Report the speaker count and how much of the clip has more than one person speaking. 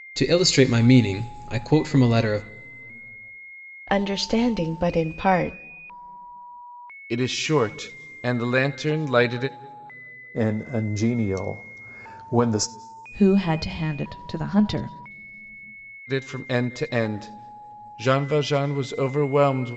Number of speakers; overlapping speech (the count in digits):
5, no overlap